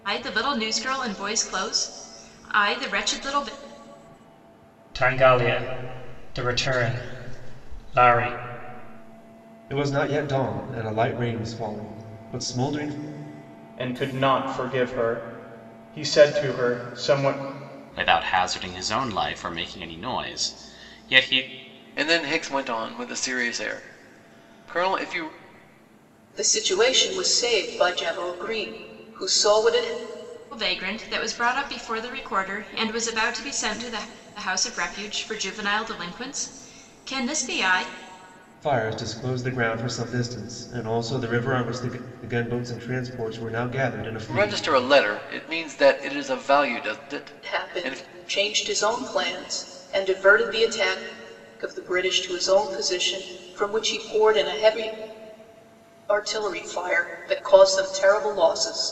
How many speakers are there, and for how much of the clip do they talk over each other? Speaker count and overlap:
7, about 2%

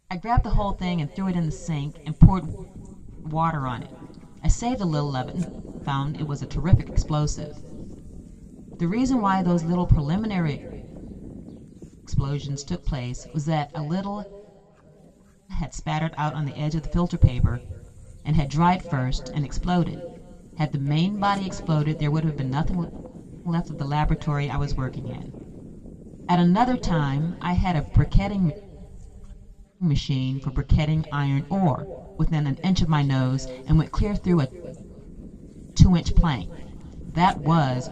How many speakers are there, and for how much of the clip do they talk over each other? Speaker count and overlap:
1, no overlap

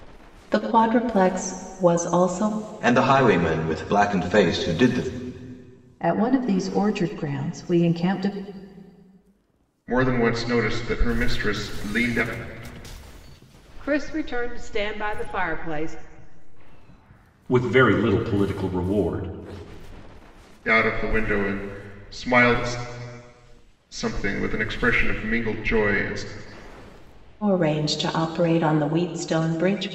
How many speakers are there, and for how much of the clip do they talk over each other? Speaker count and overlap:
6, no overlap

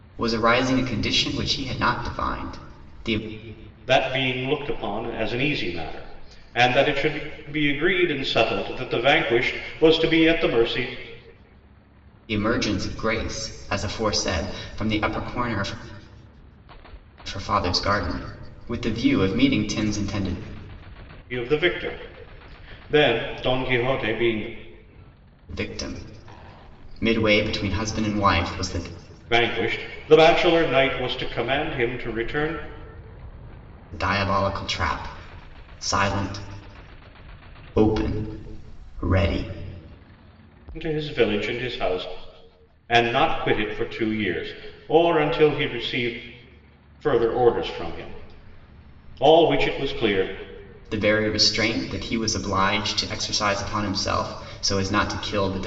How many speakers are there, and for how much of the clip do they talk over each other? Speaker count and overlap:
2, no overlap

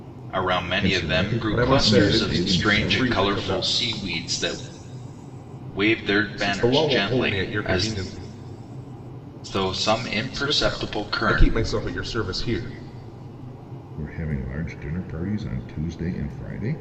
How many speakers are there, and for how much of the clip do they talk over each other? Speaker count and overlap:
3, about 34%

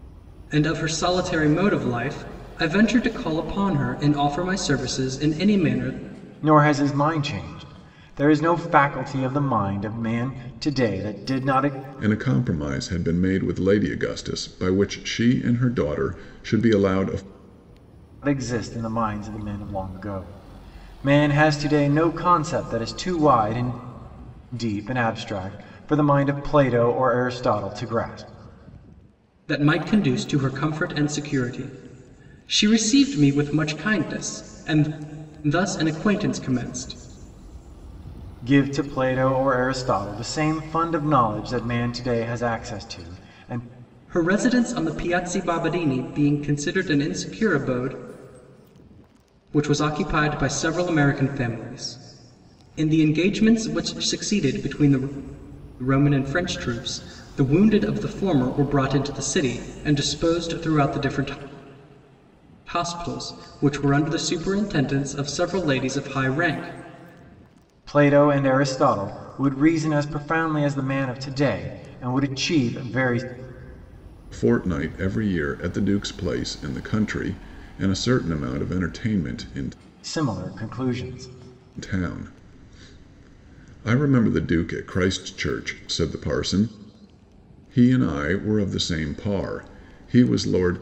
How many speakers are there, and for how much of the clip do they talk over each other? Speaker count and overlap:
3, no overlap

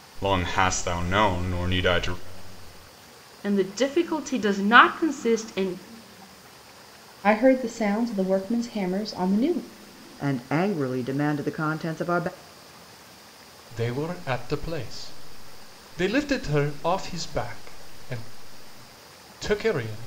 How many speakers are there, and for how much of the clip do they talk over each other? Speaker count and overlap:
5, no overlap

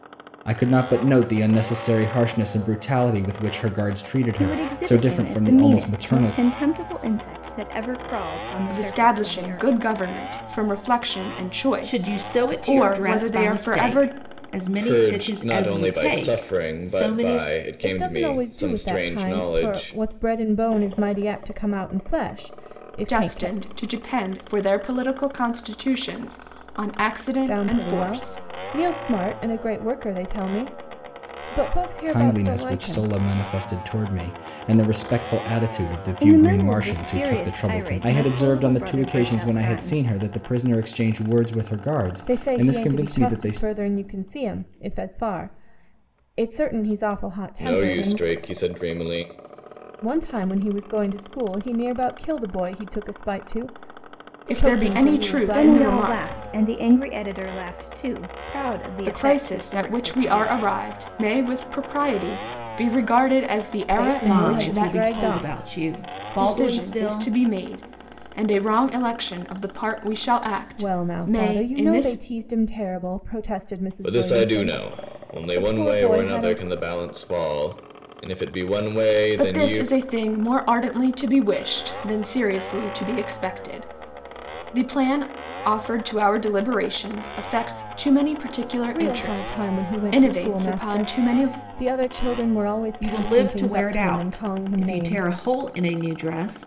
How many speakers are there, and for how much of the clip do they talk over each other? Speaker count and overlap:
6, about 37%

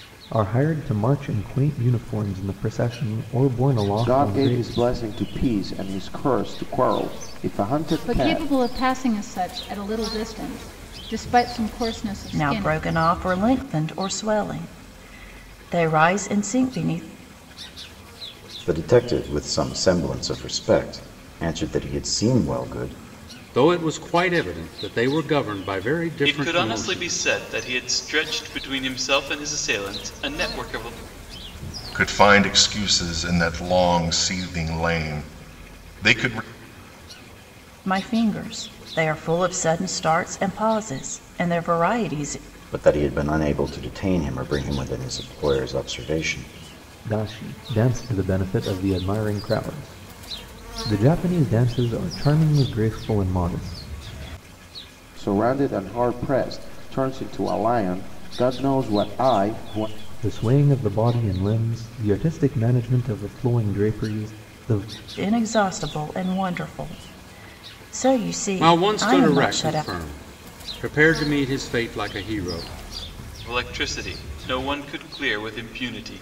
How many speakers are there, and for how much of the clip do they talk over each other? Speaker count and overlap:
8, about 5%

